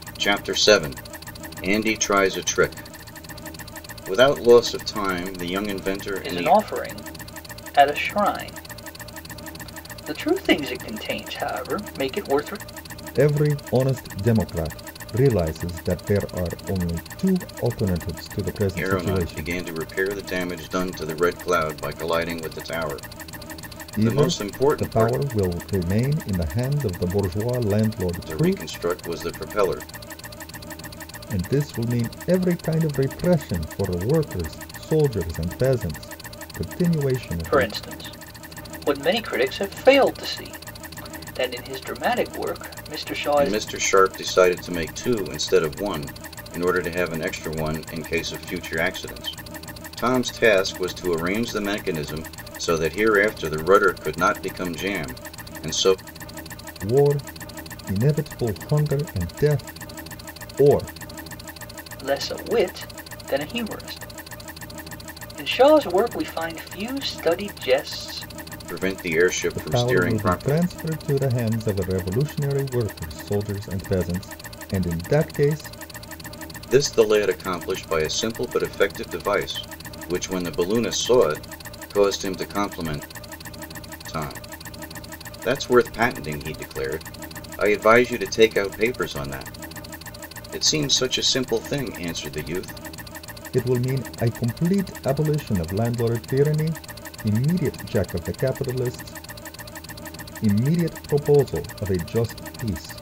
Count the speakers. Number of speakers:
3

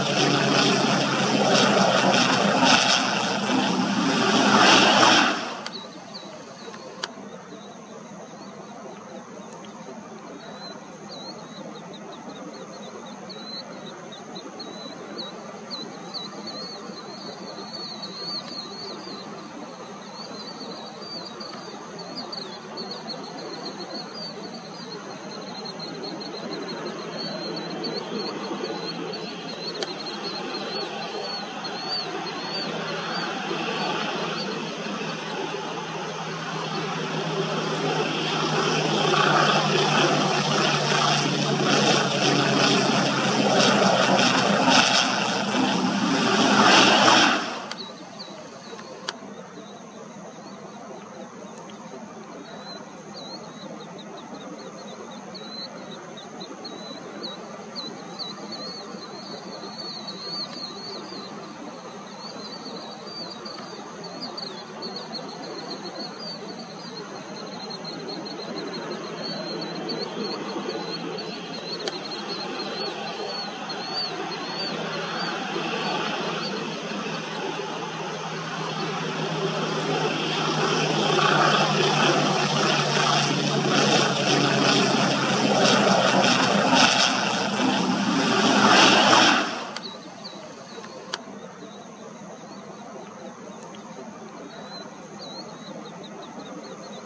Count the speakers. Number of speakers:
0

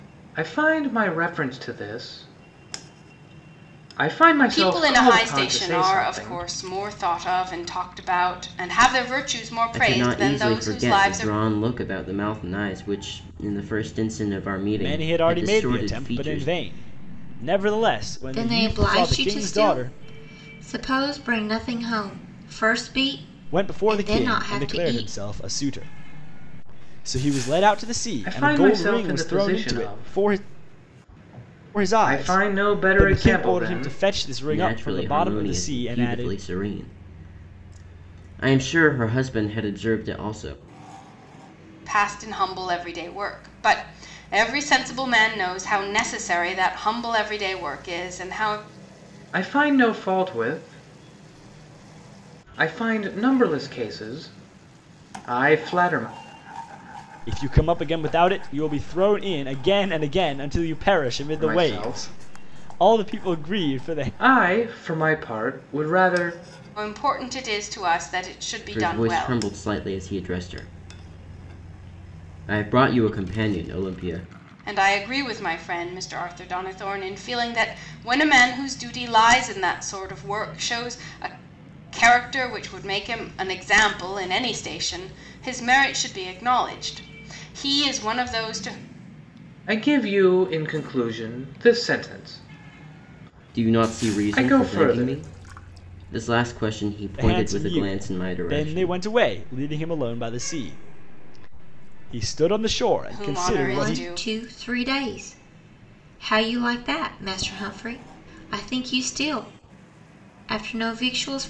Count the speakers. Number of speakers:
5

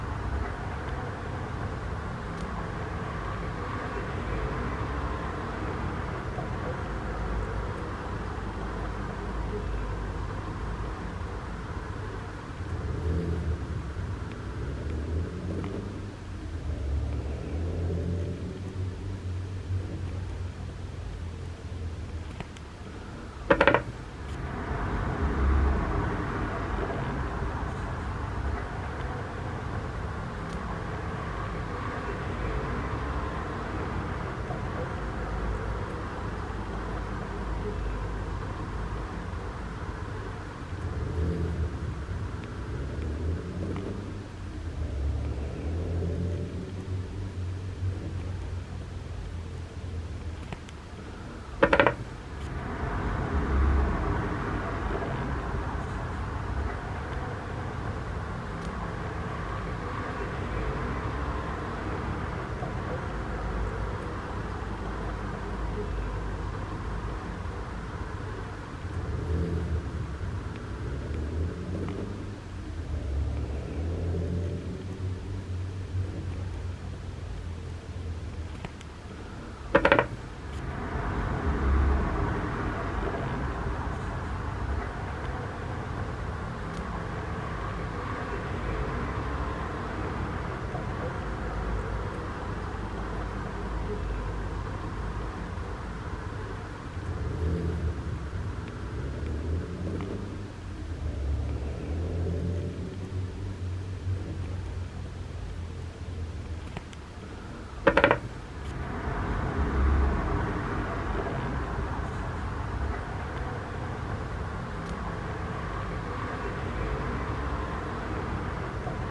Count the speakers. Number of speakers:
0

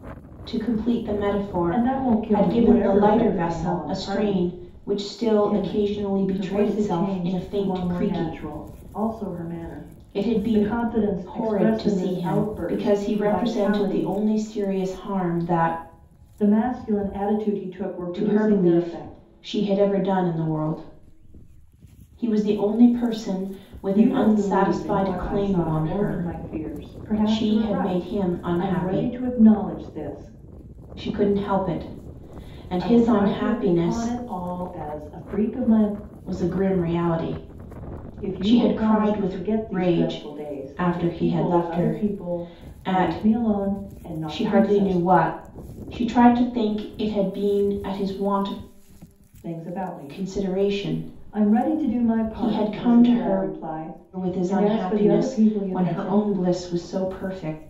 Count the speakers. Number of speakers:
2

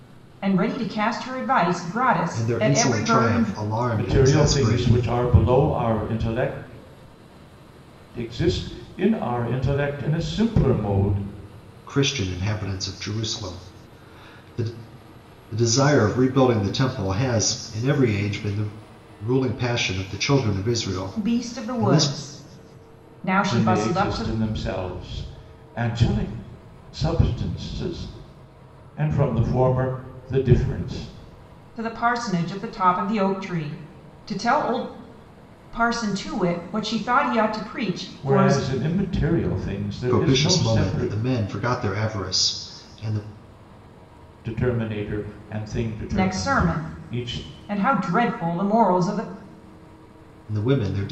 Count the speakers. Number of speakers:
3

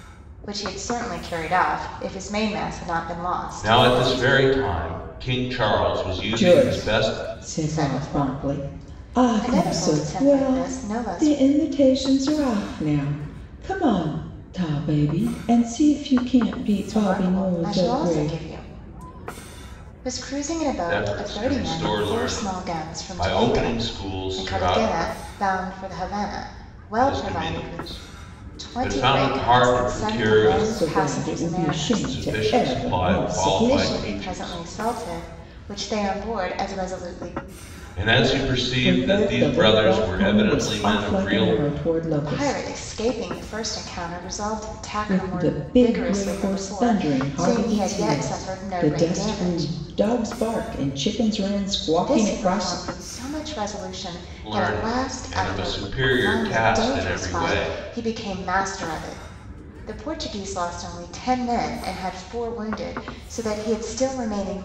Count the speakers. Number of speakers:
3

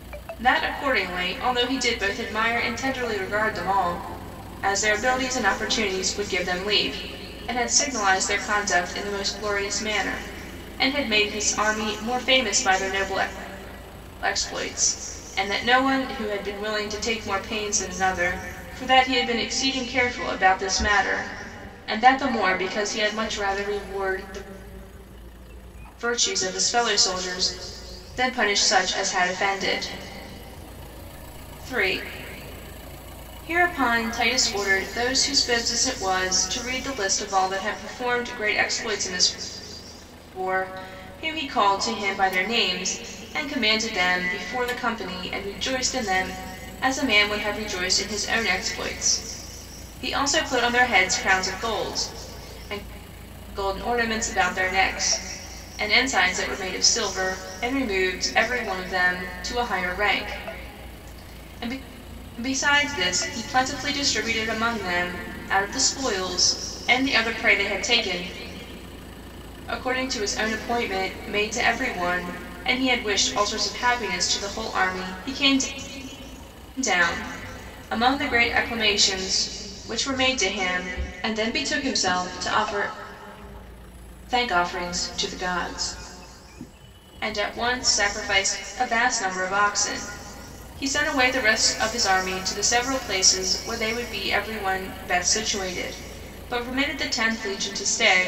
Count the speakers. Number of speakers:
1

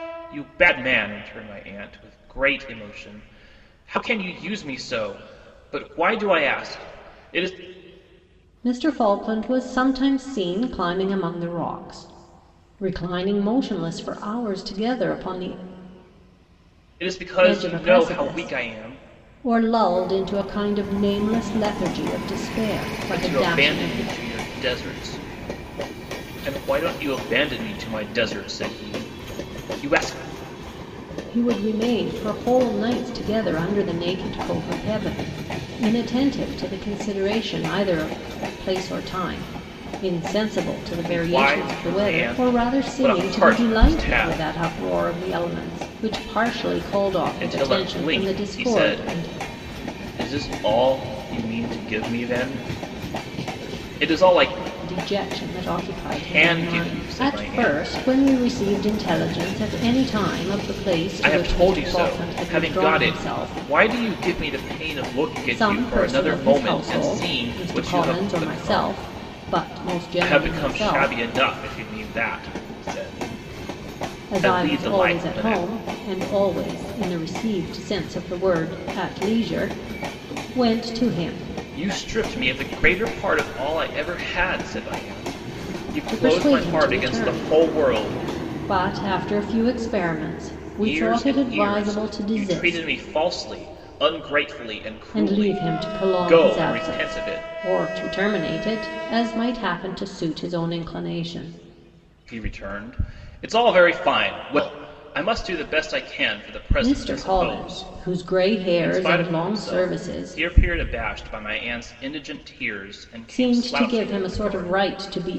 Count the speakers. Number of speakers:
2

